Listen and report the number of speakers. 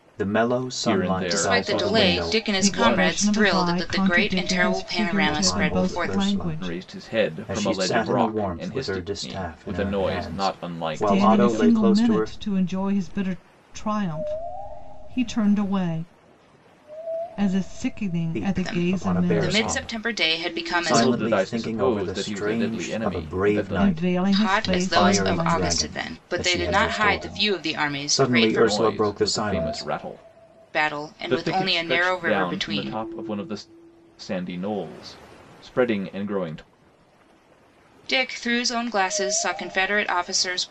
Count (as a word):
four